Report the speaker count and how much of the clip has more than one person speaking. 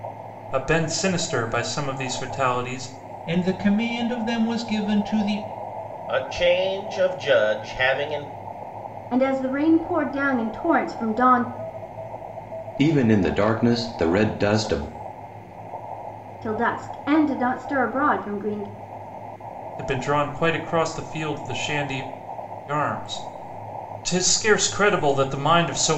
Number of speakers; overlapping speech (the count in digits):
5, no overlap